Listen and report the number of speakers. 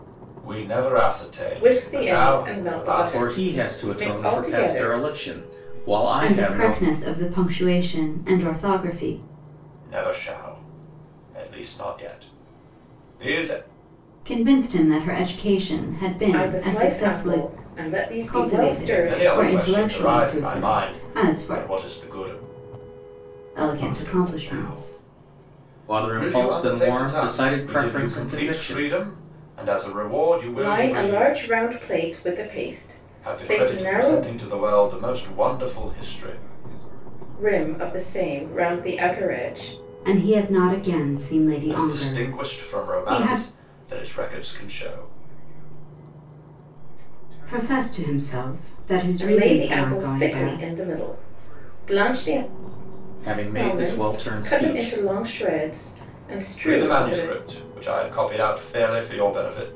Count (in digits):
5